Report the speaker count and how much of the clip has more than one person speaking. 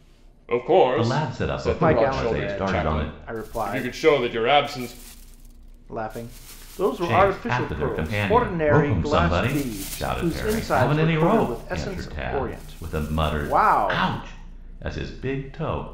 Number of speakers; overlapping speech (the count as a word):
three, about 63%